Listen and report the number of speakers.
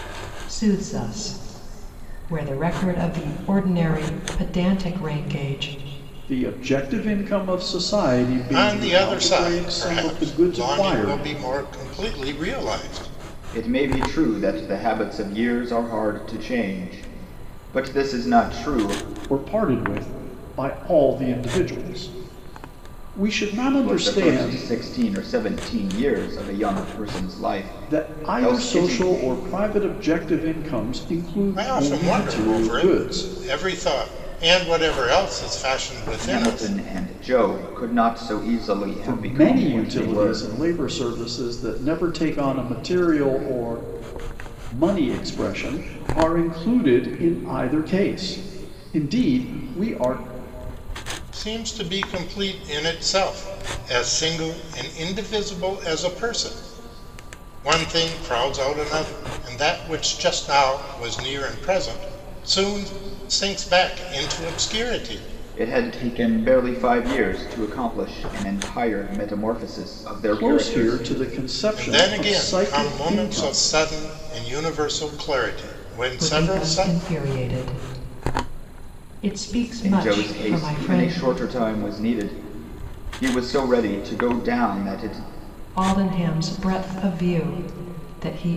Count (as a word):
four